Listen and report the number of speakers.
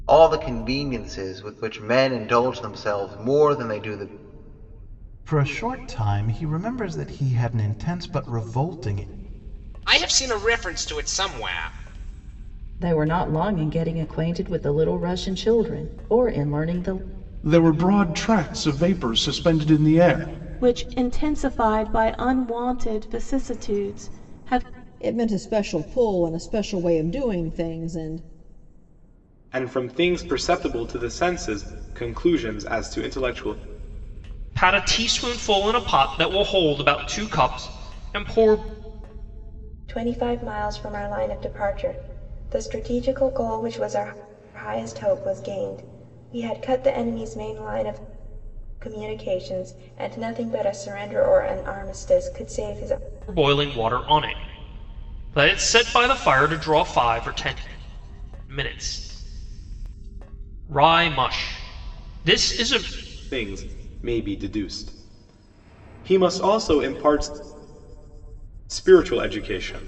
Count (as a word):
ten